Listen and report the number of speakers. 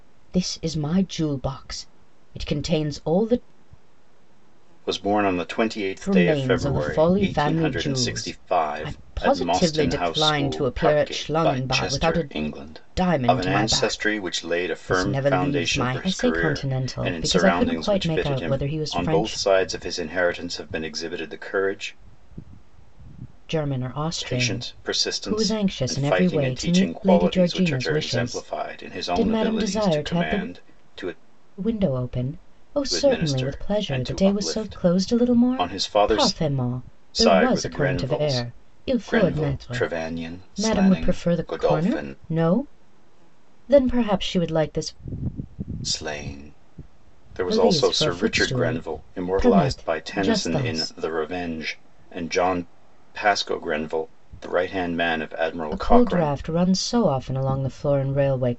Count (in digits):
2